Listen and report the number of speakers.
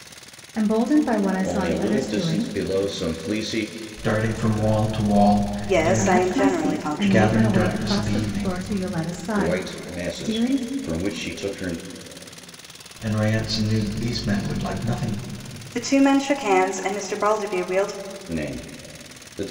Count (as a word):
four